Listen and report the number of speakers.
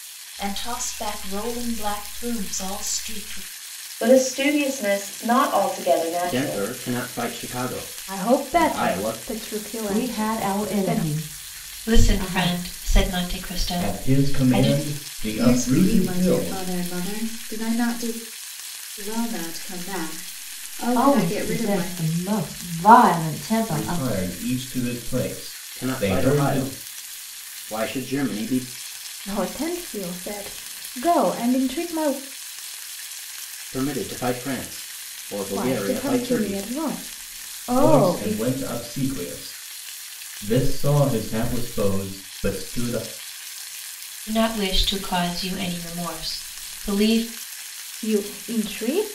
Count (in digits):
8